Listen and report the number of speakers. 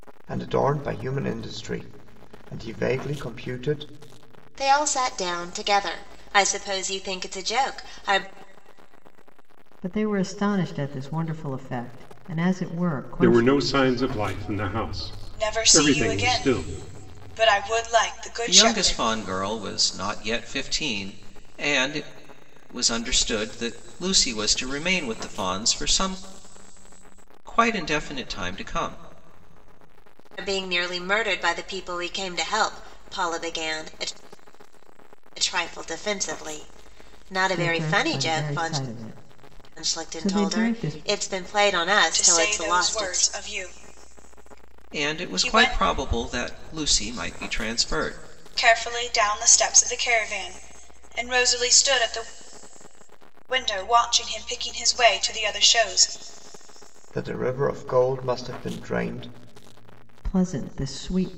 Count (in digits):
6